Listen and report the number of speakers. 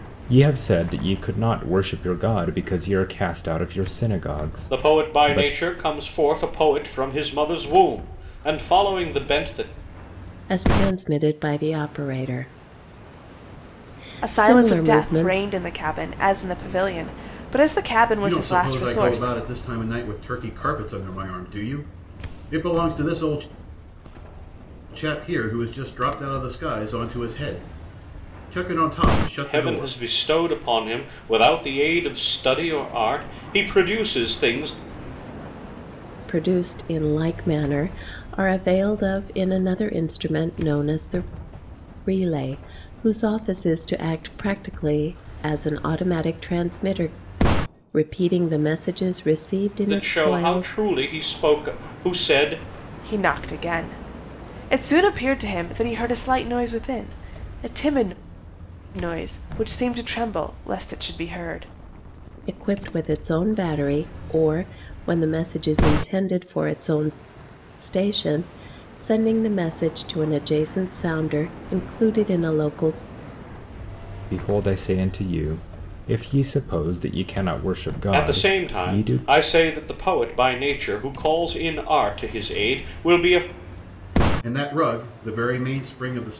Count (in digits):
5